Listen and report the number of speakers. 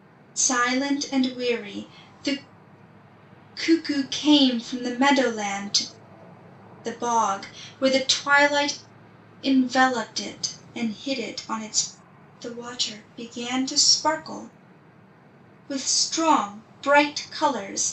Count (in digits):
1